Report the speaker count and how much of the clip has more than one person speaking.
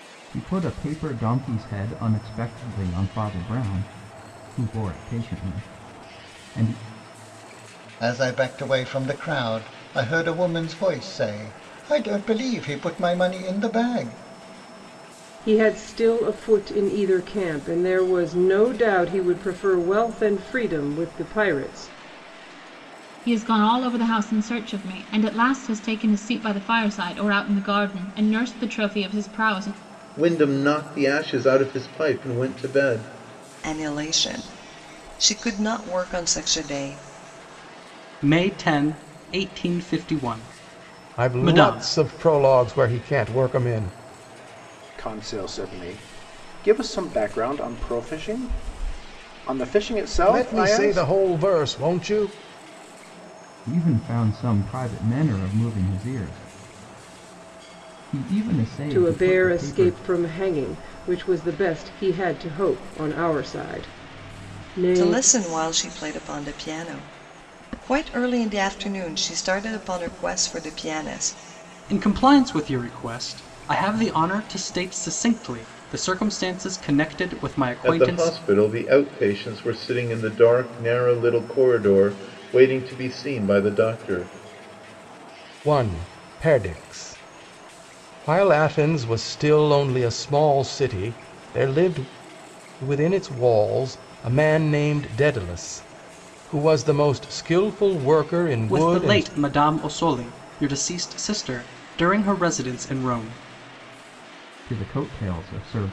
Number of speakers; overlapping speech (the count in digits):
9, about 4%